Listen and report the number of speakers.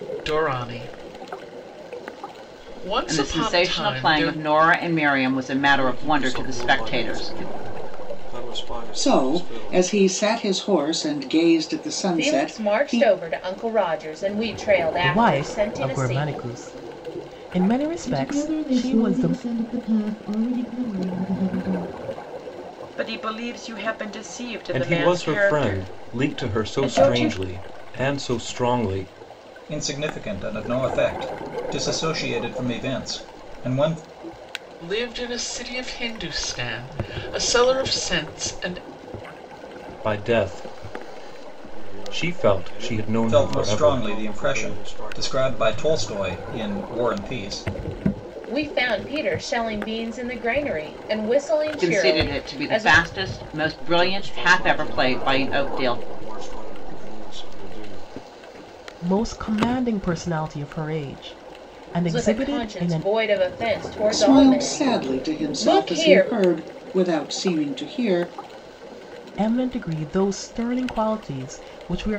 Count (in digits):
10